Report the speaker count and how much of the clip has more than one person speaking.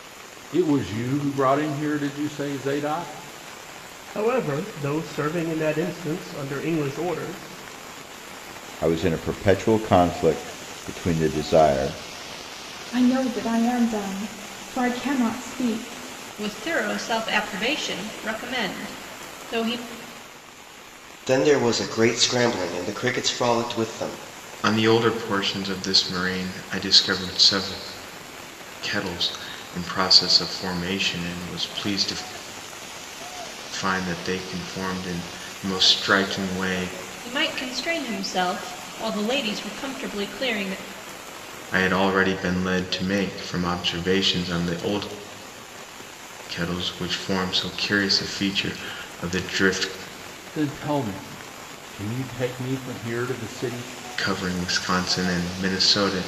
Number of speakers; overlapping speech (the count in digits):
7, no overlap